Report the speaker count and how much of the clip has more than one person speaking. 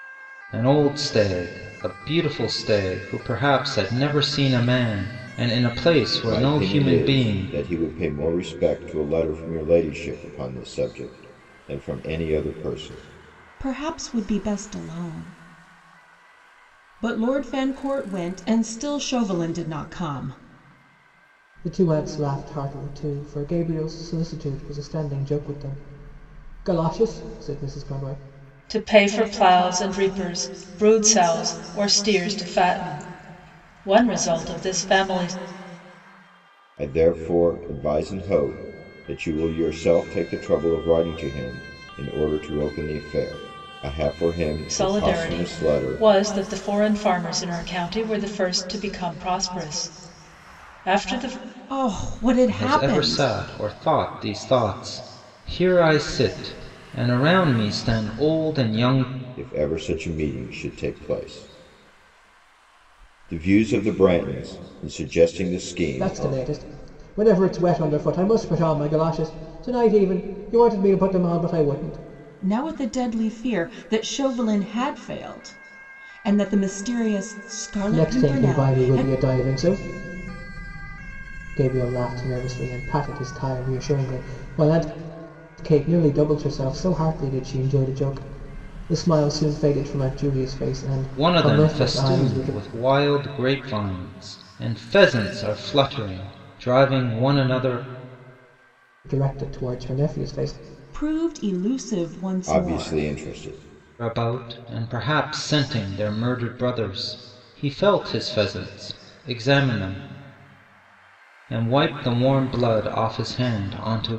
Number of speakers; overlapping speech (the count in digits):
5, about 6%